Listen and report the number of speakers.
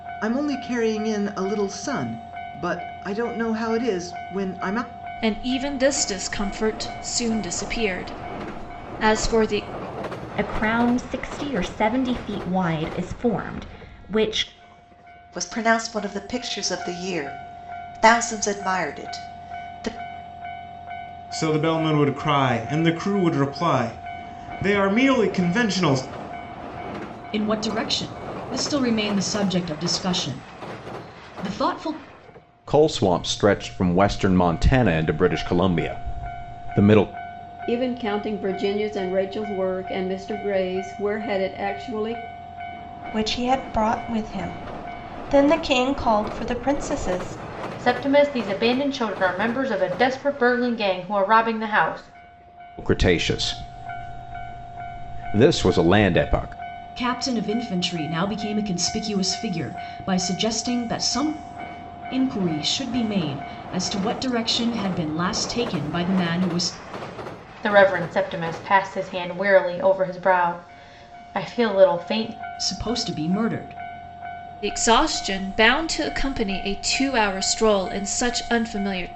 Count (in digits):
10